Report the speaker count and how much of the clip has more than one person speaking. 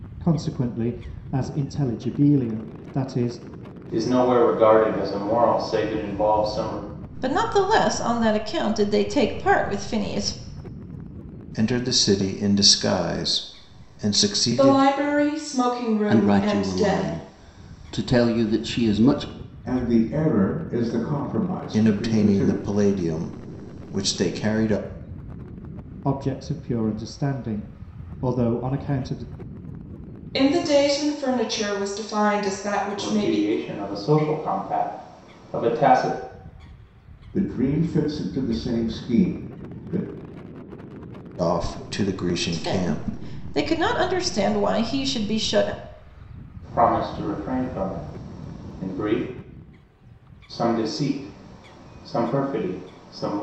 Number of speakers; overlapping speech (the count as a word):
seven, about 7%